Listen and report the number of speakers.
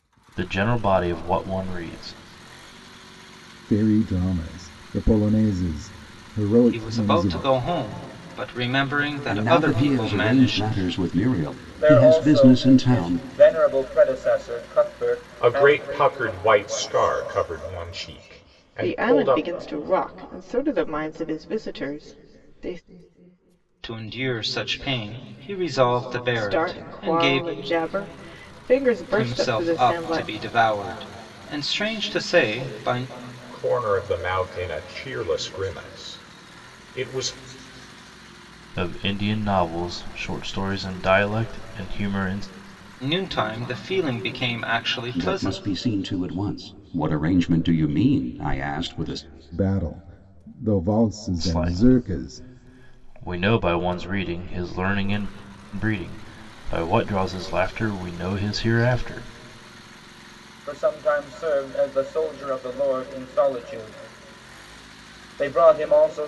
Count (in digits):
7